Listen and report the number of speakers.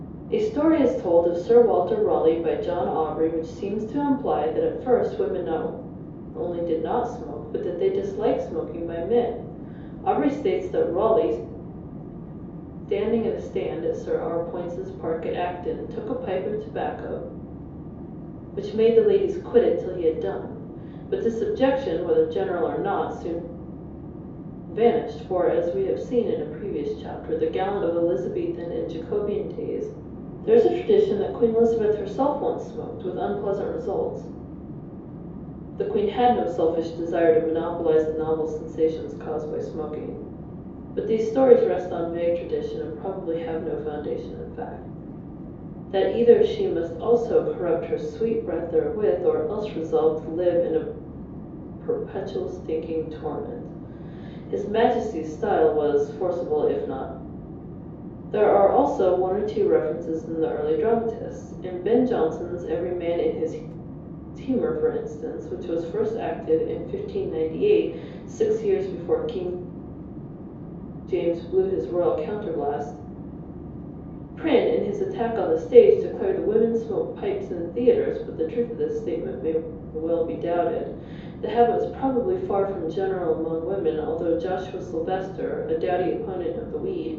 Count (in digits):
1